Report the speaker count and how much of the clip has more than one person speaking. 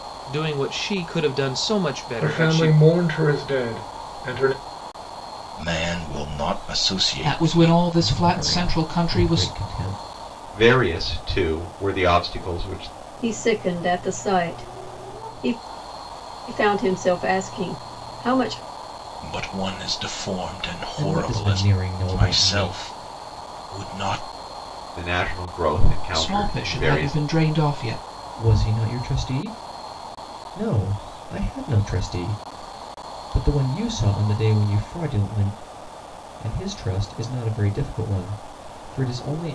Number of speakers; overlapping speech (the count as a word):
seven, about 13%